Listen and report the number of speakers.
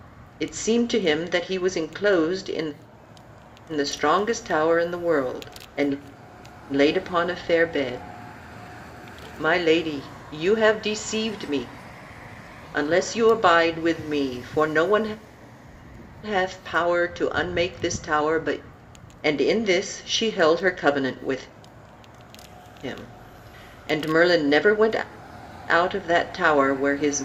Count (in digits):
1